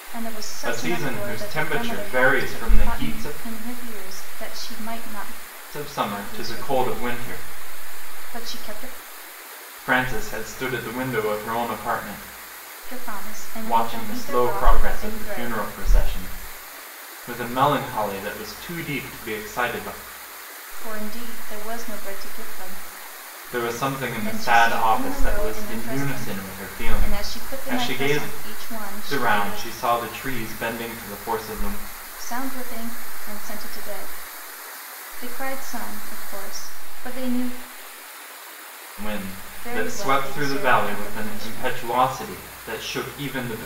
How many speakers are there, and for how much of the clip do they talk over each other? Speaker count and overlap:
2, about 28%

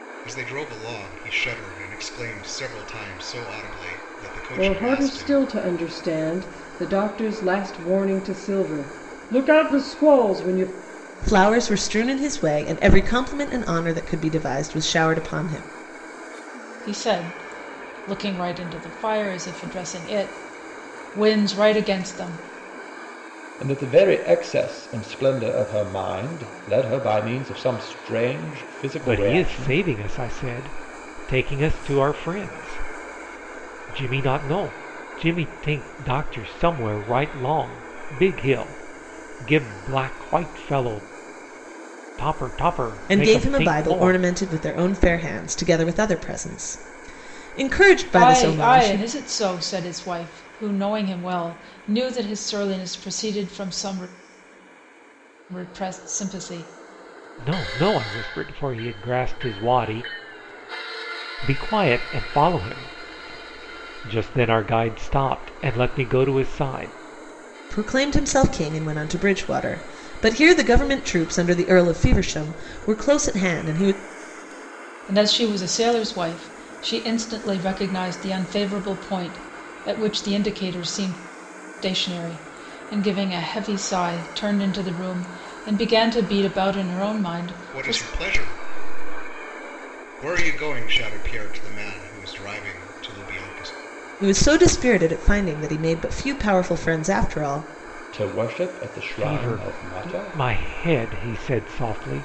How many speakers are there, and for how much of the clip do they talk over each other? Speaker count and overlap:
6, about 5%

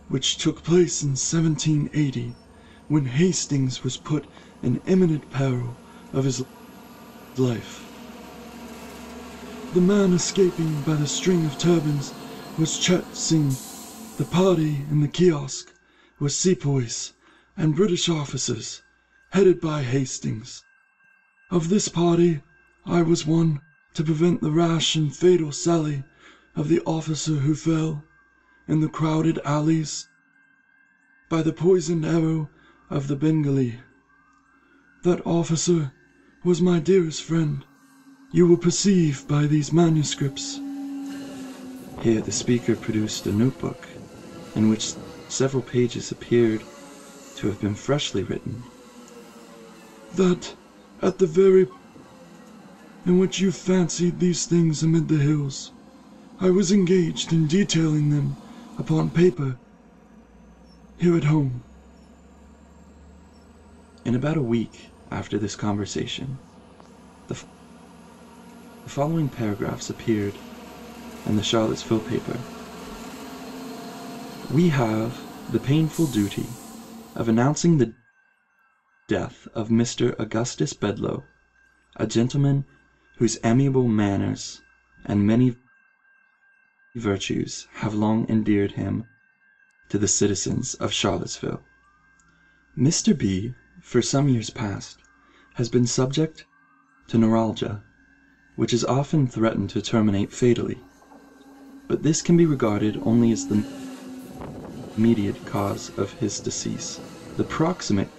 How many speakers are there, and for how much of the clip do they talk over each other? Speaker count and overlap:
1, no overlap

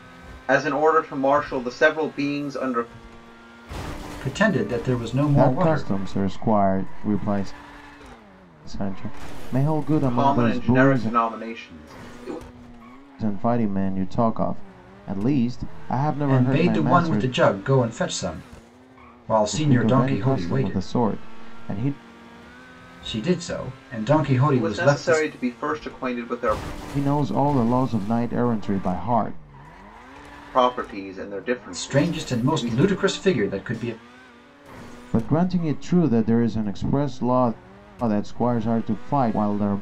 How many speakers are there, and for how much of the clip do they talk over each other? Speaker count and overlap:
3, about 15%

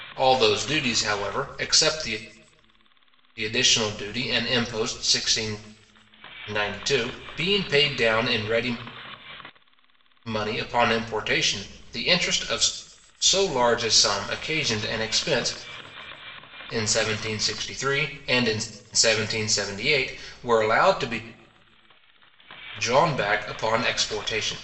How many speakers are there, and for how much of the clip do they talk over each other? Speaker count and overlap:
1, no overlap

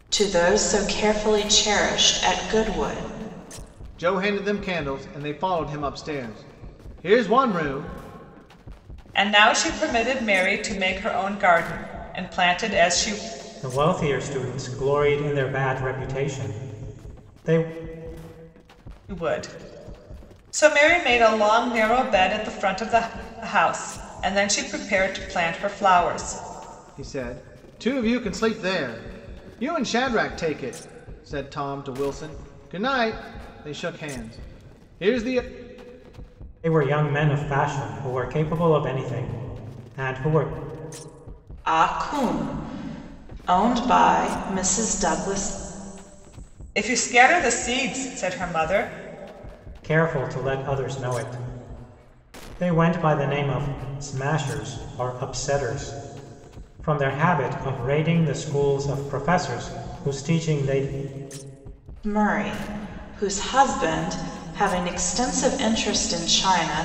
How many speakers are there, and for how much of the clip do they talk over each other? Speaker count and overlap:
4, no overlap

